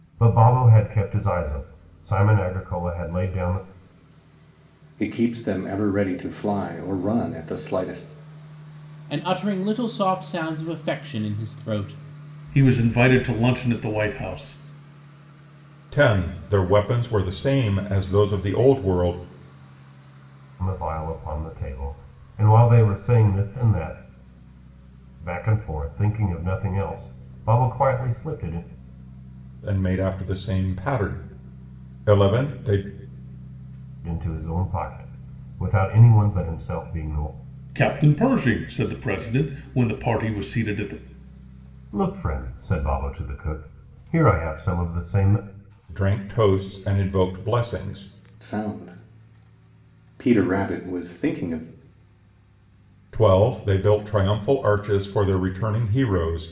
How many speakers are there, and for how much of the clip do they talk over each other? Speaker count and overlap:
5, no overlap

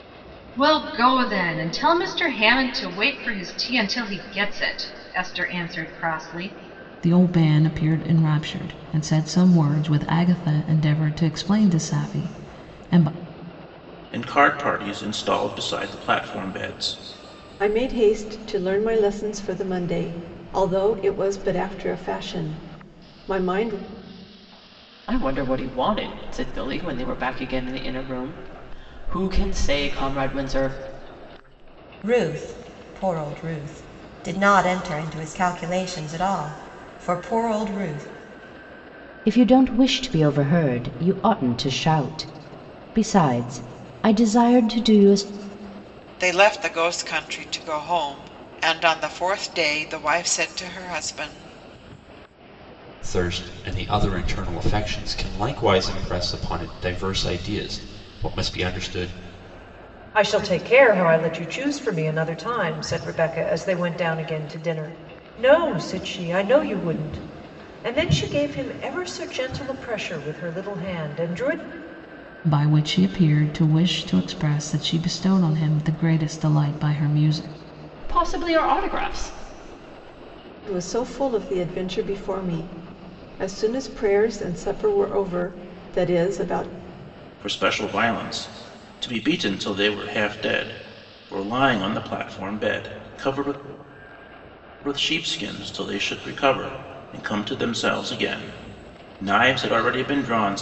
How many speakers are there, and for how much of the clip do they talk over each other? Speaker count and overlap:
10, no overlap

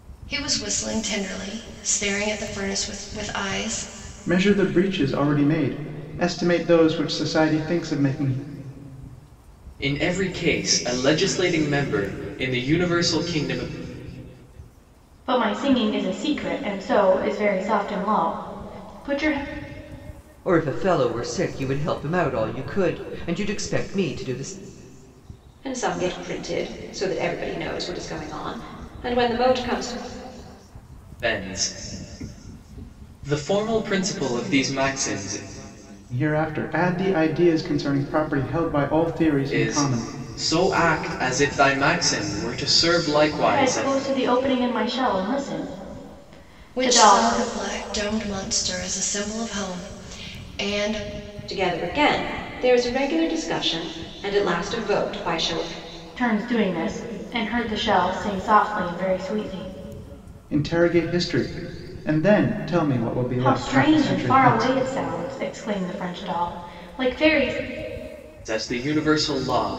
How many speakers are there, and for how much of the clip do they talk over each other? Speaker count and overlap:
6, about 5%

